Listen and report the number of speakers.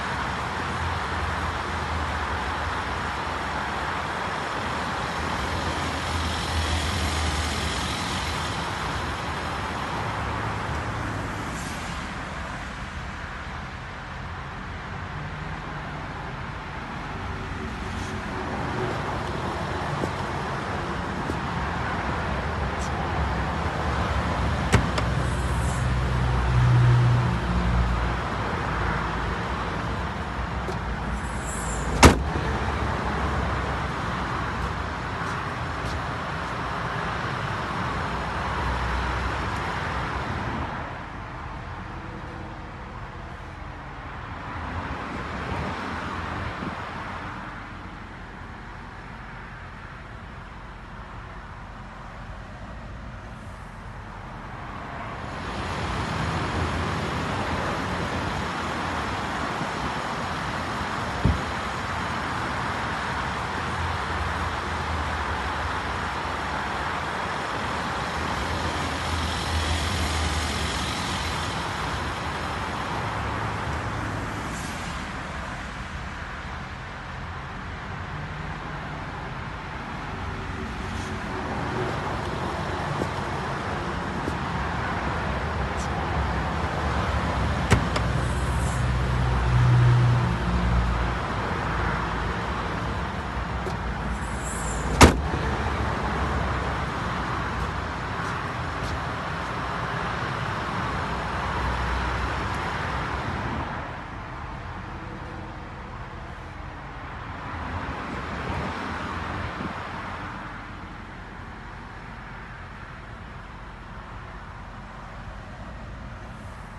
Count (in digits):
0